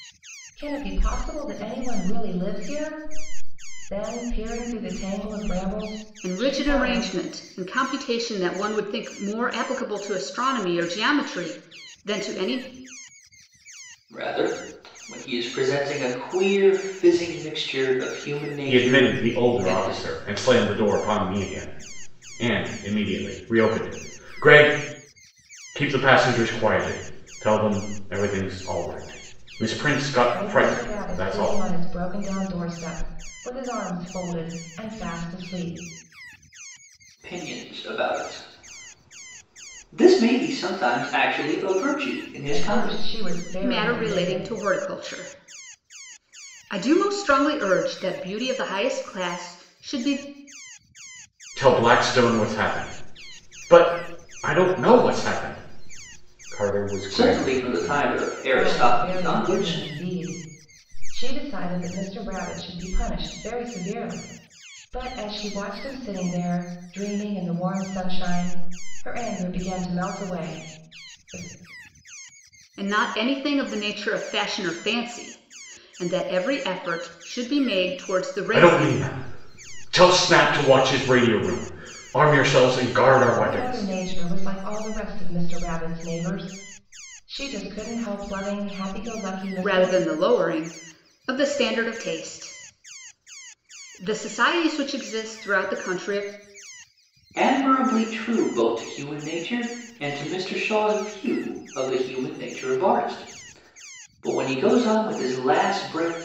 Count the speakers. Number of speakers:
four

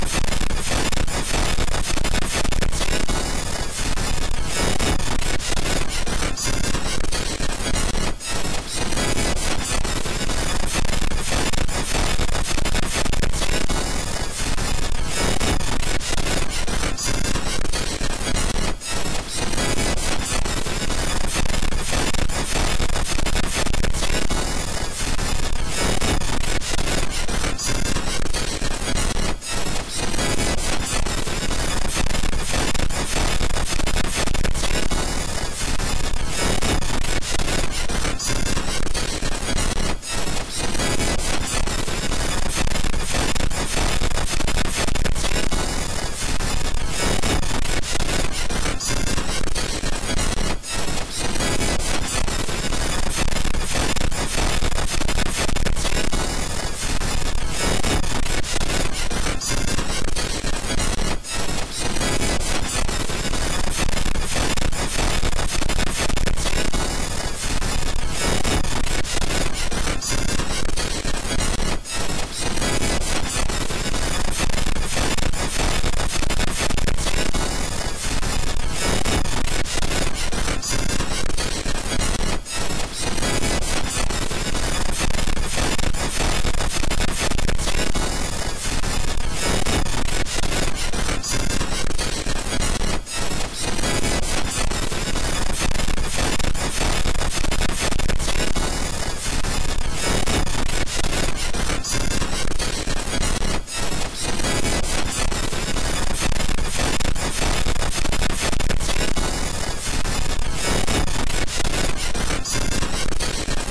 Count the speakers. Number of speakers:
zero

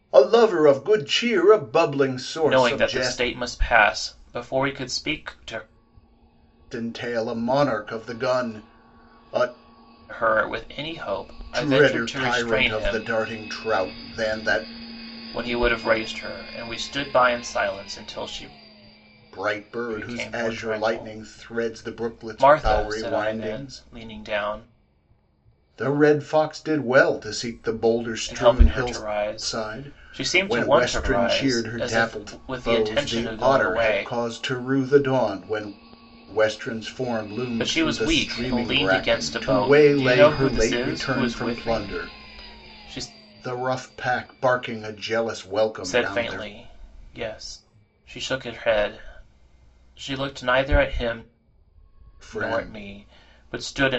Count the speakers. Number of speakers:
two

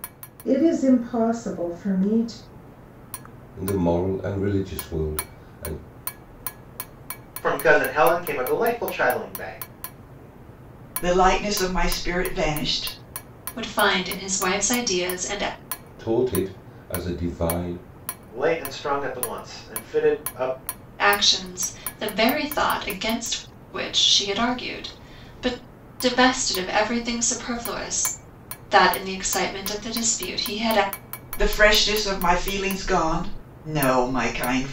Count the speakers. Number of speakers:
five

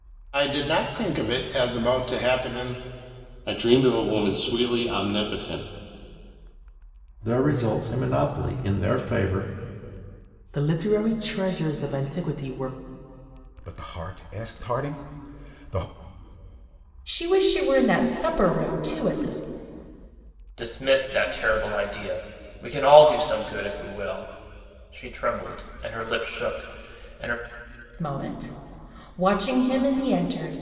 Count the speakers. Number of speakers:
seven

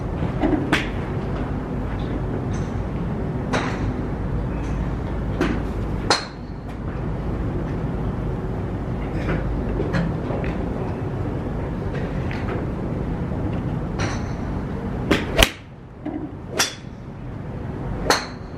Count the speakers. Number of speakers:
zero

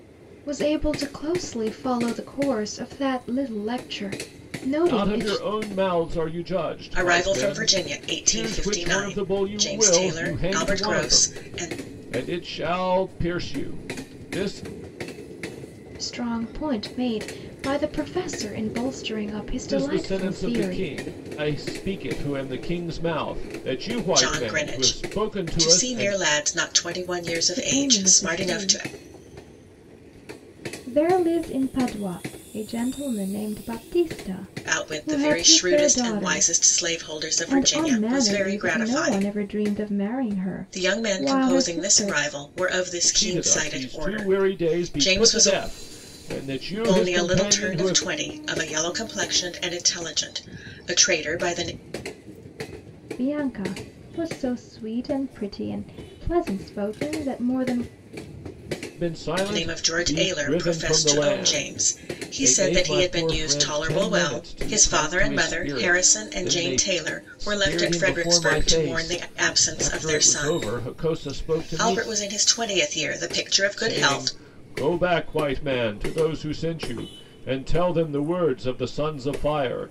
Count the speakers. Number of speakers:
three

